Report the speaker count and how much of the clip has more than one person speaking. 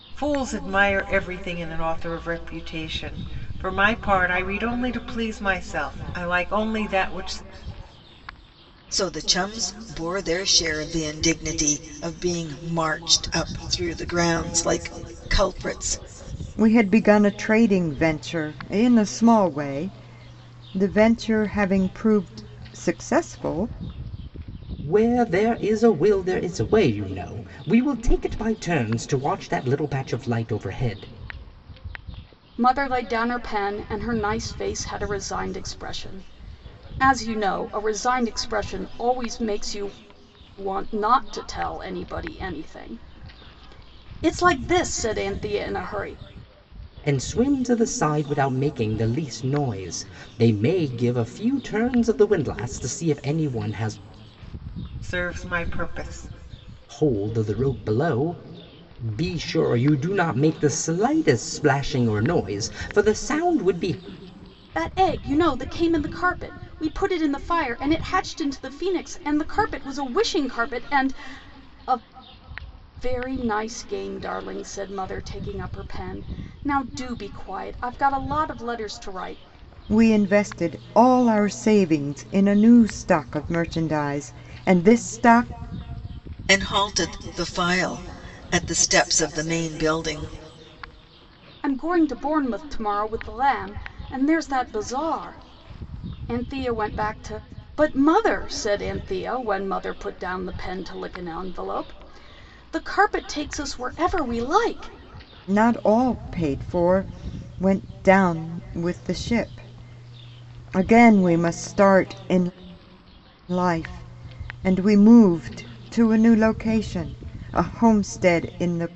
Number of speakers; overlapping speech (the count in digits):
5, no overlap